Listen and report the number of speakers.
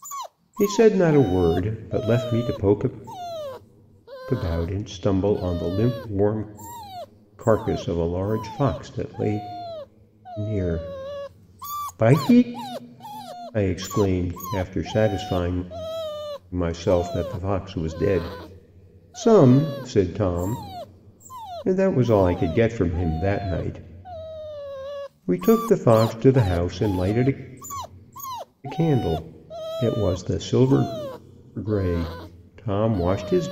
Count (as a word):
one